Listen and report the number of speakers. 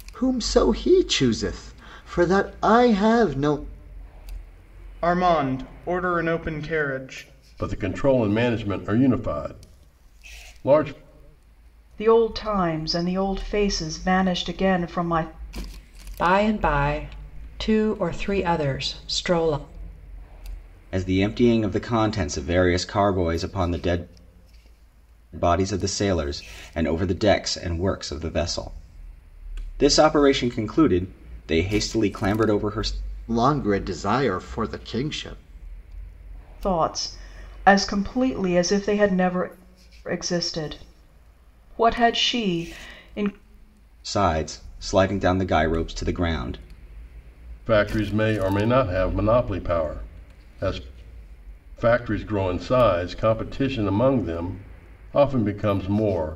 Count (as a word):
six